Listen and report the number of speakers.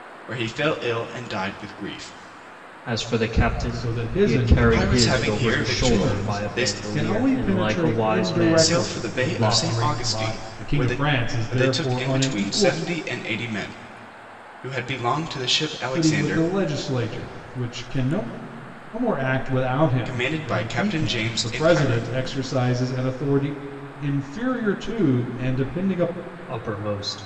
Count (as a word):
three